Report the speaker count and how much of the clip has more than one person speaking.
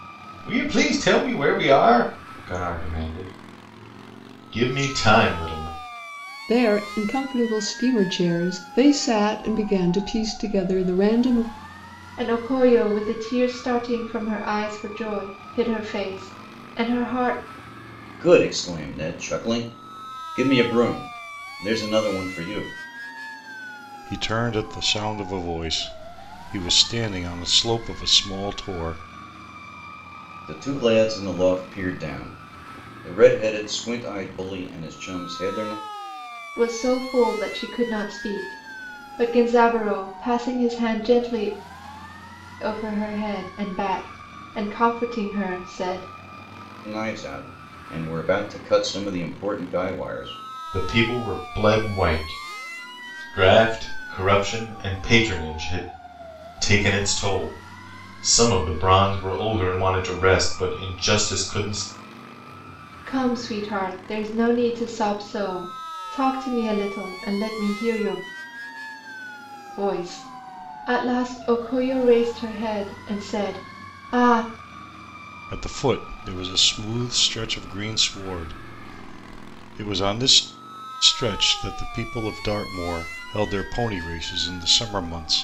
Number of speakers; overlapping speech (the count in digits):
5, no overlap